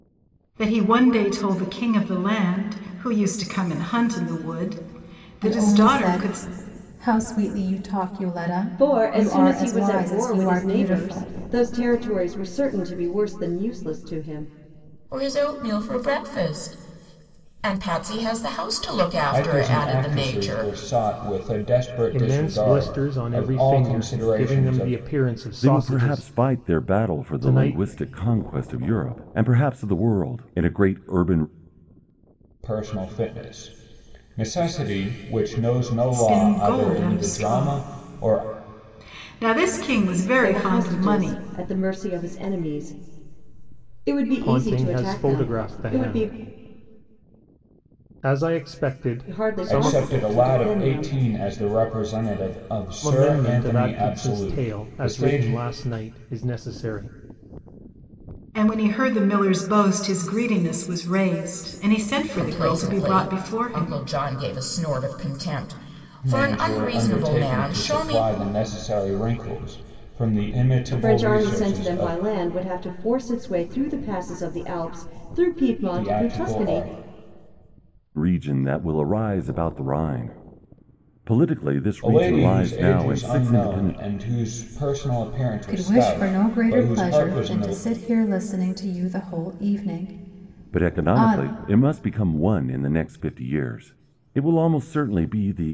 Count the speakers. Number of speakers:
7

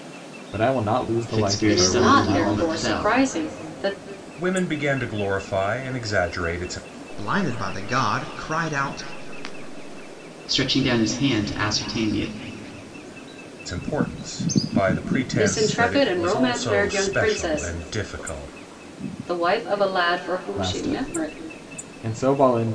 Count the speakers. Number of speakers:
5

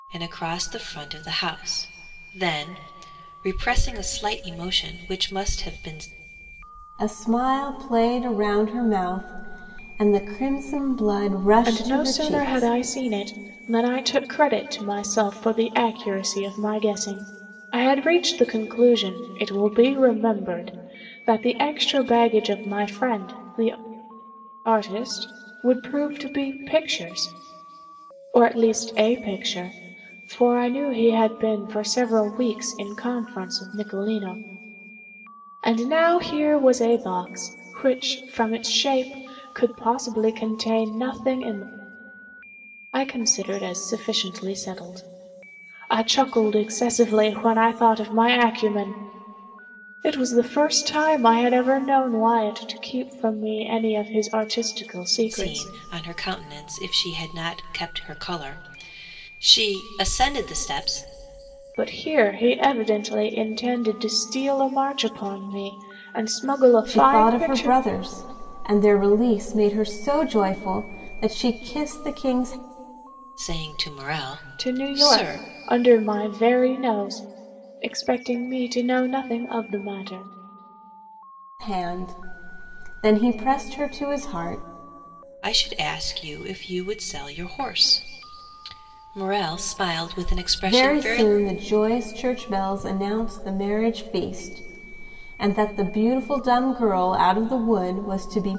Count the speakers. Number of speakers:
3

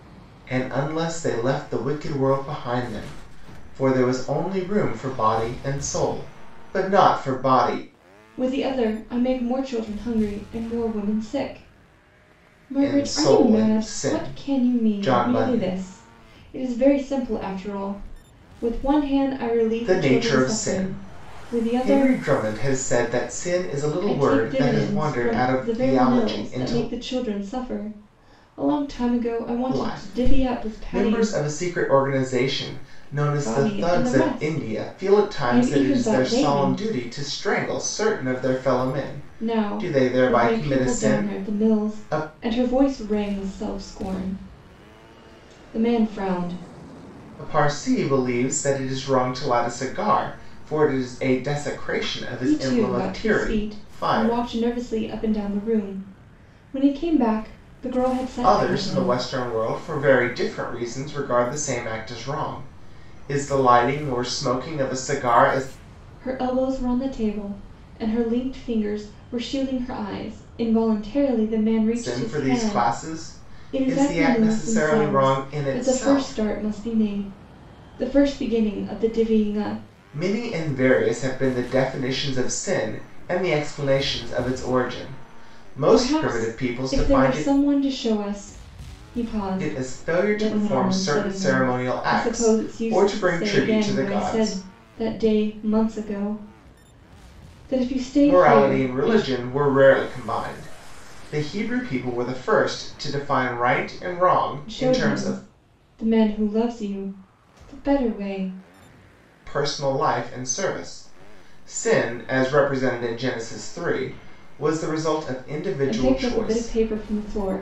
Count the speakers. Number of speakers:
2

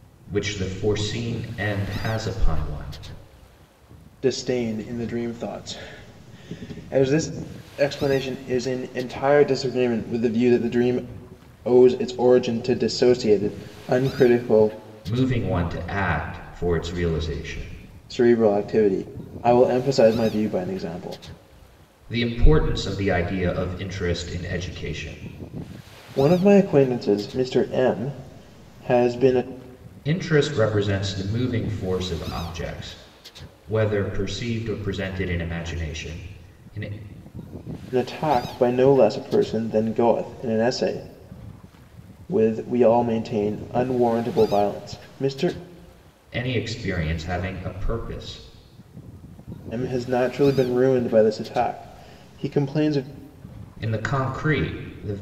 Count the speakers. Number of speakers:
2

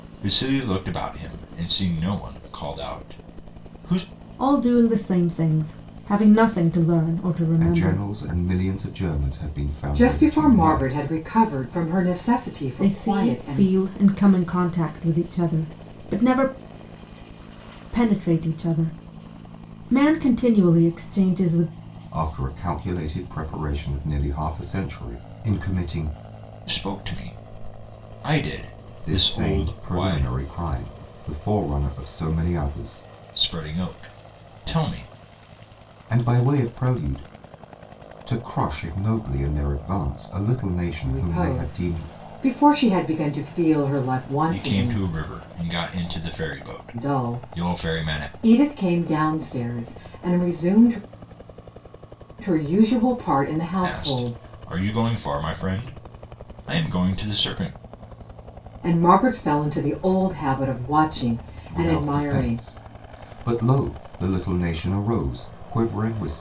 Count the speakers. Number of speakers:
4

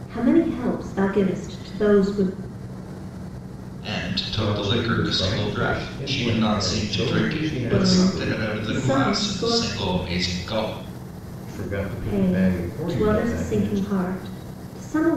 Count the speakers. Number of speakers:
3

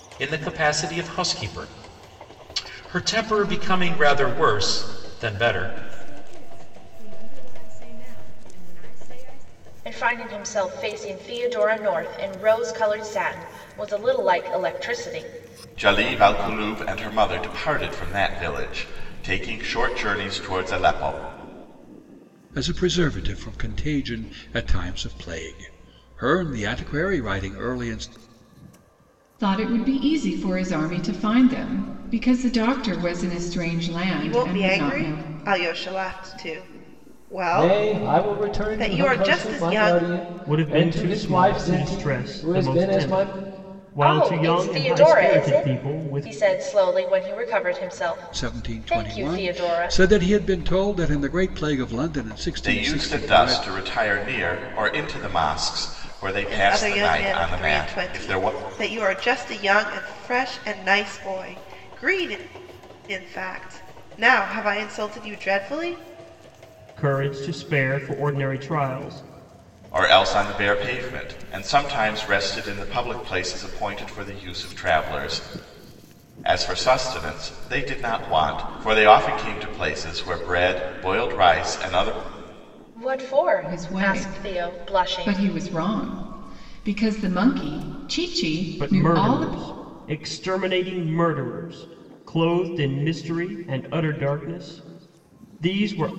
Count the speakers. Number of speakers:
9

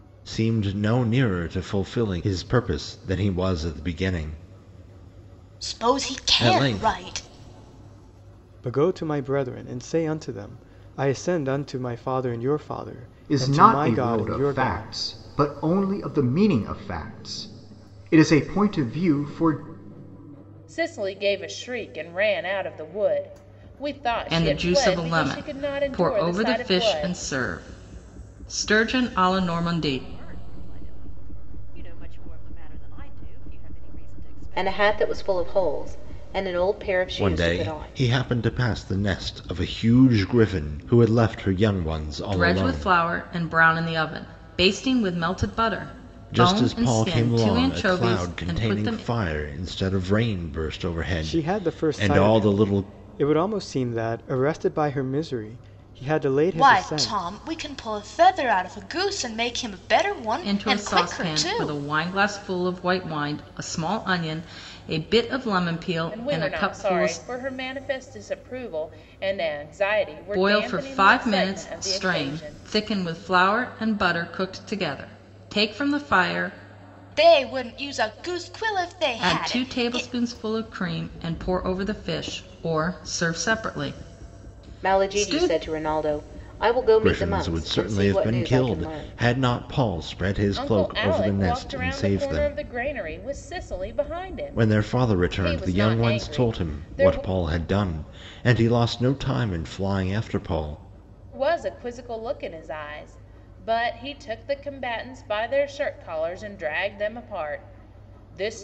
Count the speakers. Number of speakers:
8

